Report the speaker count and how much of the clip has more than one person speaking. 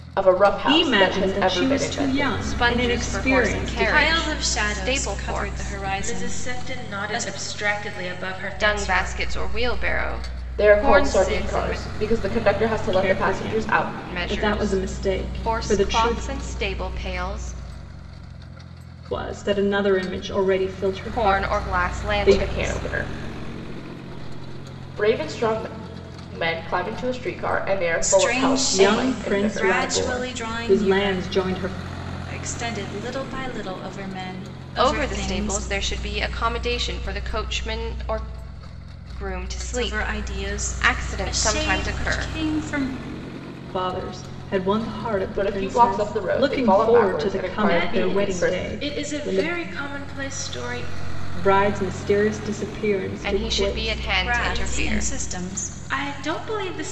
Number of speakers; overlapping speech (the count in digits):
5, about 47%